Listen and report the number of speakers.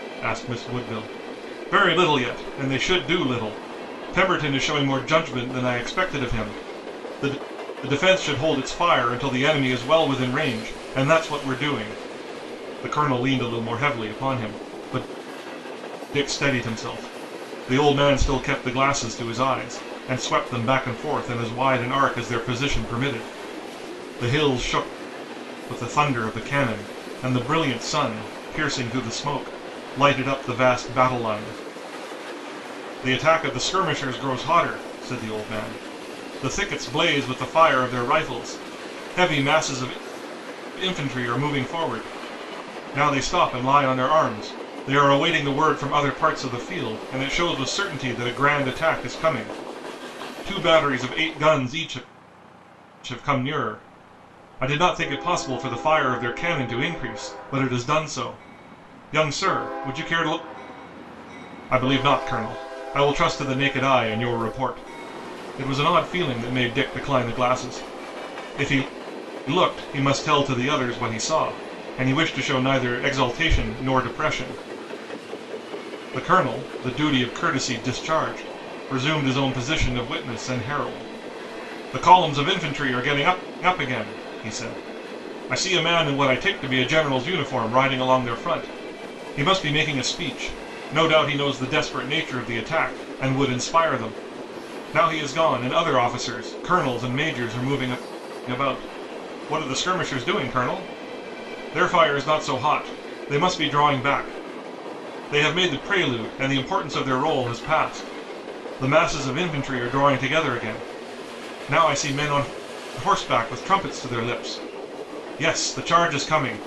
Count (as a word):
one